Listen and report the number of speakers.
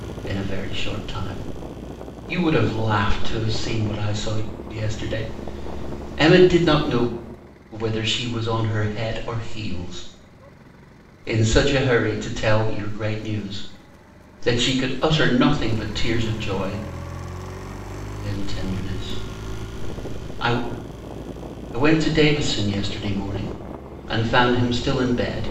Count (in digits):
1